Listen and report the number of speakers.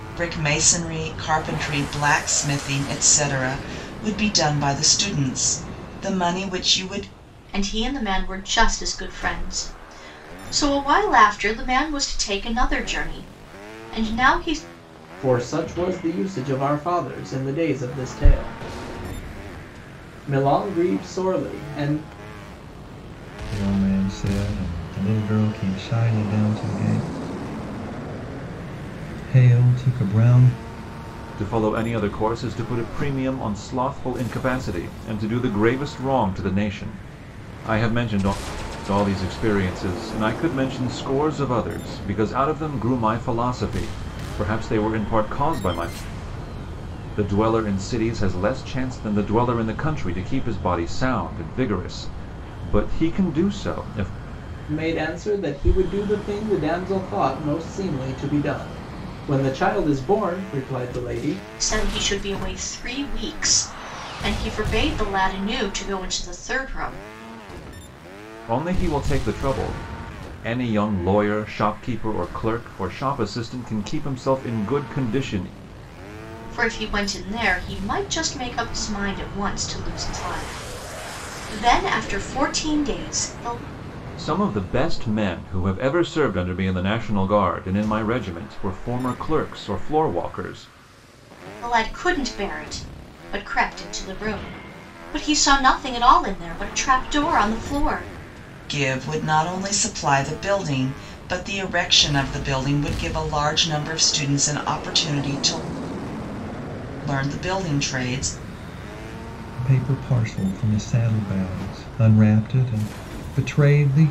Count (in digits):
5